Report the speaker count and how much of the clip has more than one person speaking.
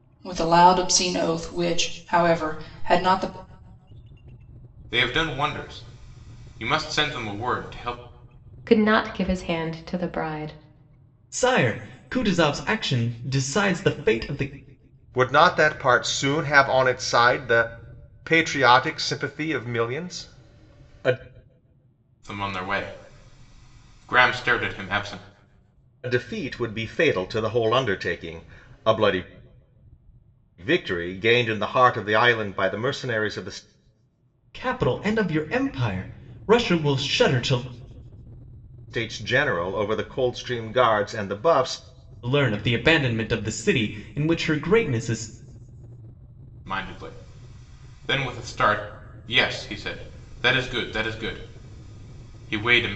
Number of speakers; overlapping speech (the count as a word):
five, no overlap